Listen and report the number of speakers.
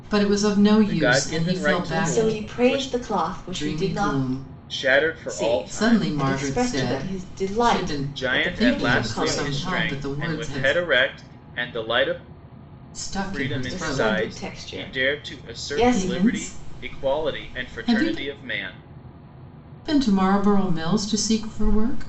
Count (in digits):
3